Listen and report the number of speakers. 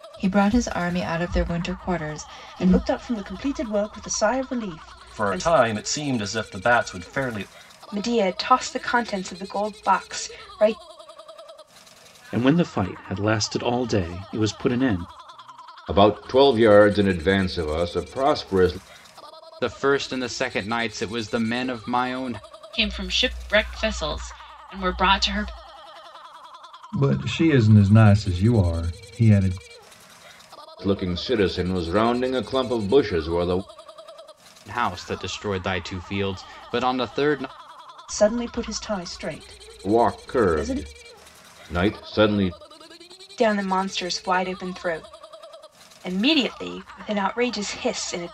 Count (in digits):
9